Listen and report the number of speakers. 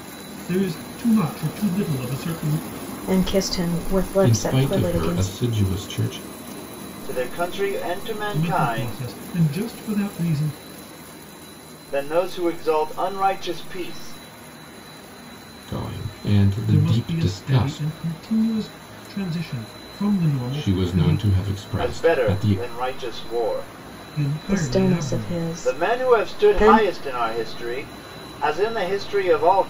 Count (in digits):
4